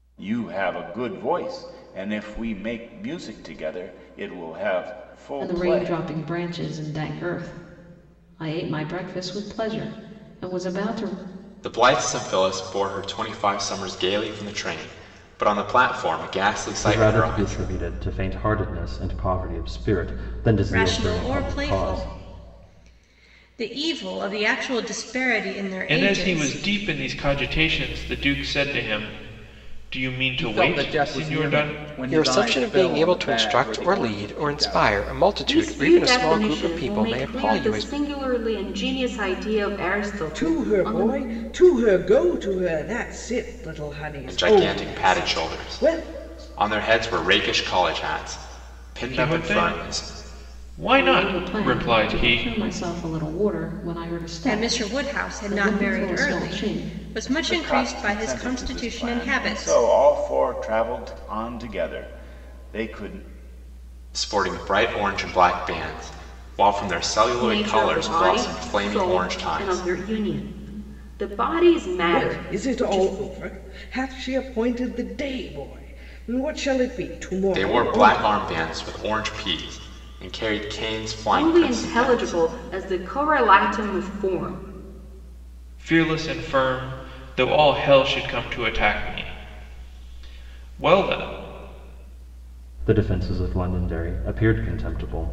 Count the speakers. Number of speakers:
ten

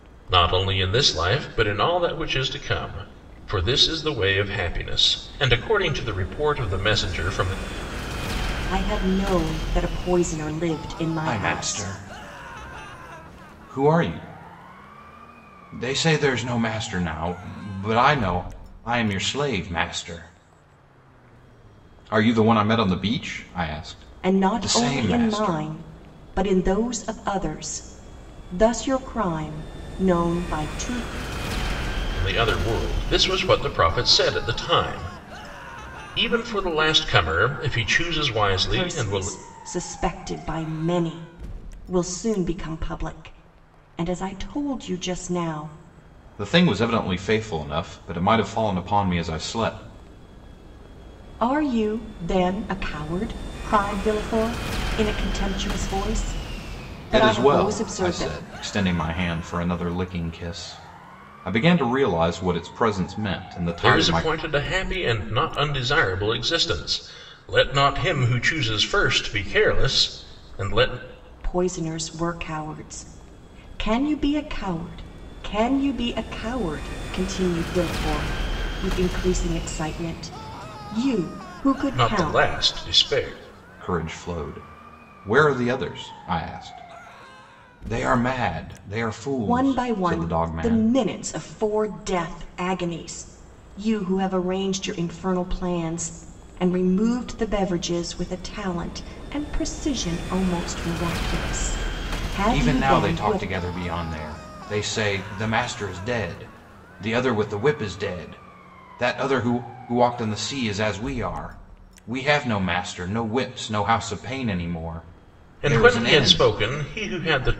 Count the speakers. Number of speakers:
three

